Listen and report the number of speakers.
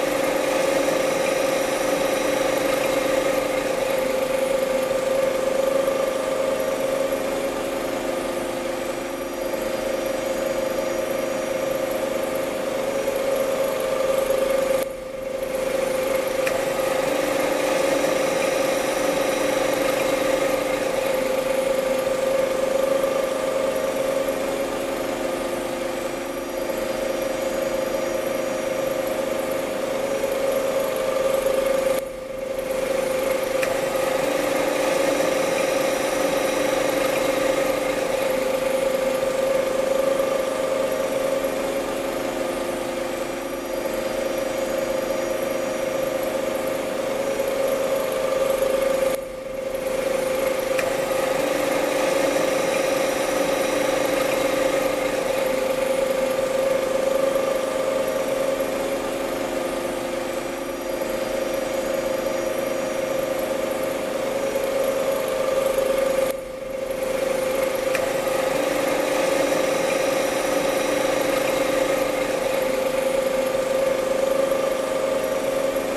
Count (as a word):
zero